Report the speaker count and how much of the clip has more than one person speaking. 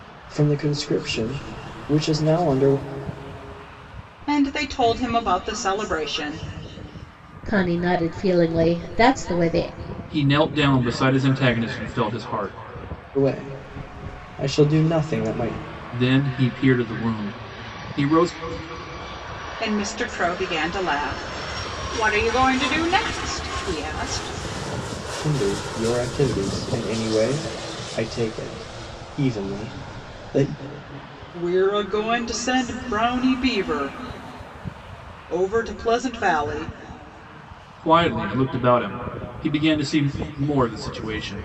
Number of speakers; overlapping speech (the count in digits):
4, no overlap